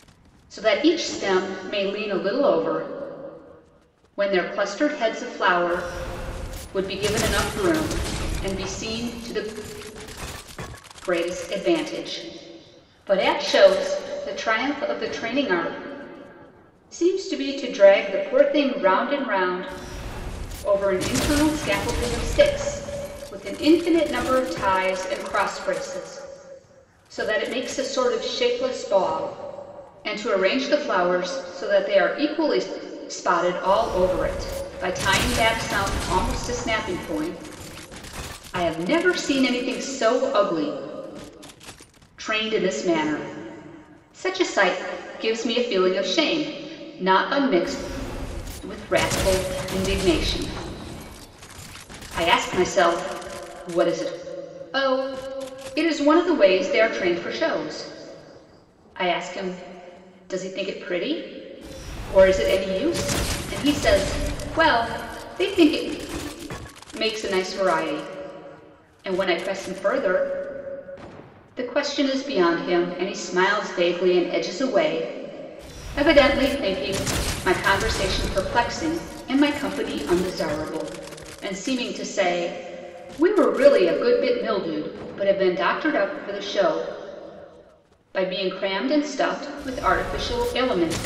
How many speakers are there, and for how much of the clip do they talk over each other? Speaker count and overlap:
one, no overlap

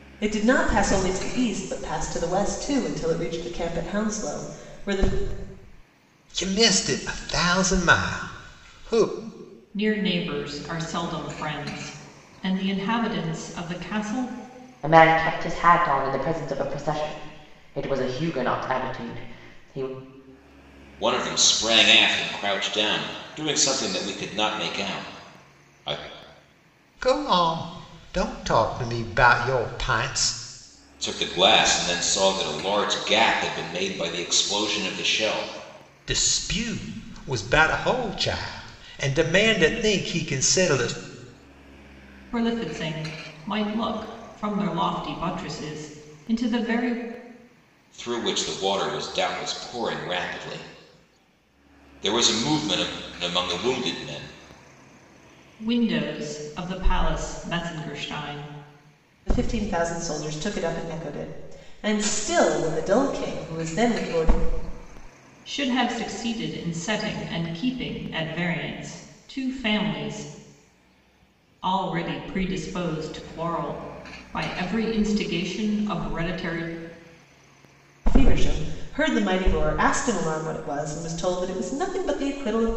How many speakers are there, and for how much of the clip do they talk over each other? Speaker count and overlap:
five, no overlap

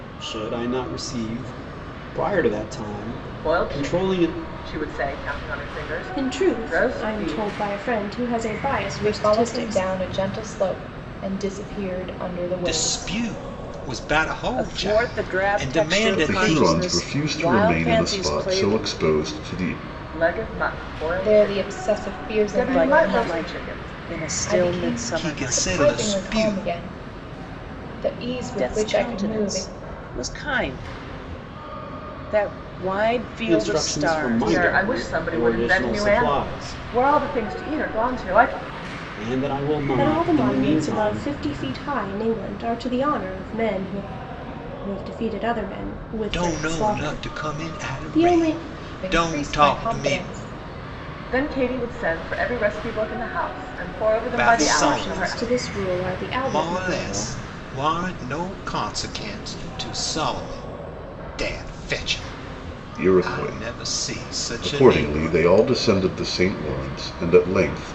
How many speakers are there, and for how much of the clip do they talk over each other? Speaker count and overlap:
seven, about 41%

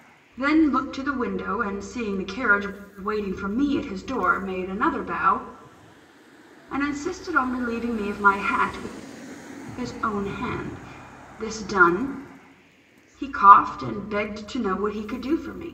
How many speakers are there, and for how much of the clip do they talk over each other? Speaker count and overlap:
one, no overlap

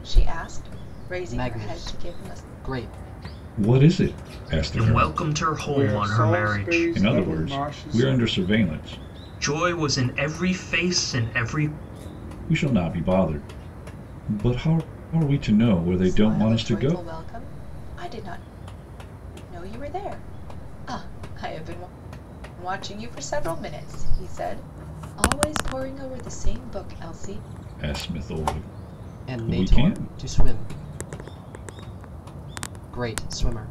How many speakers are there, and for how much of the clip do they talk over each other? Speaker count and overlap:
five, about 17%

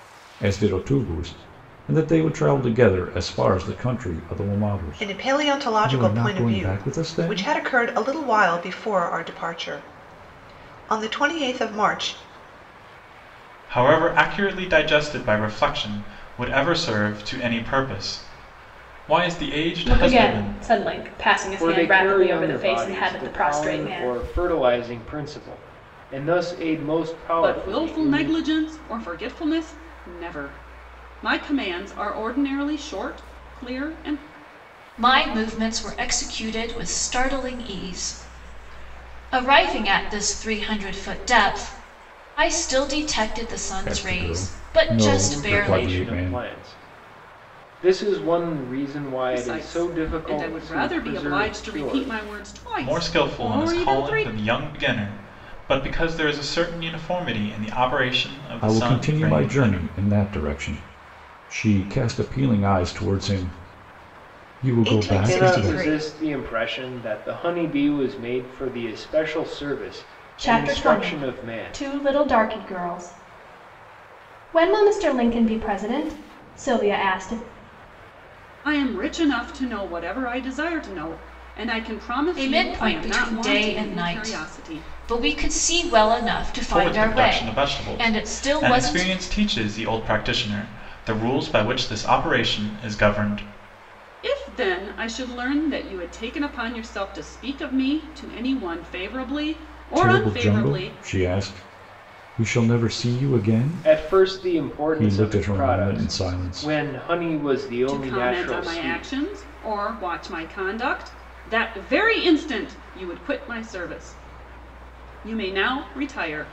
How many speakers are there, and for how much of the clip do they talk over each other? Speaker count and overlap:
seven, about 24%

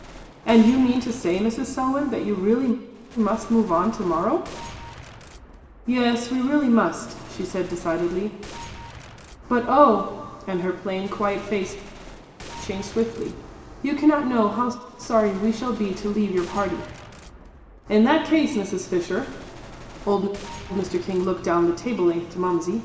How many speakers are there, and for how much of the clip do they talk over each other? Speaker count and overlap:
one, no overlap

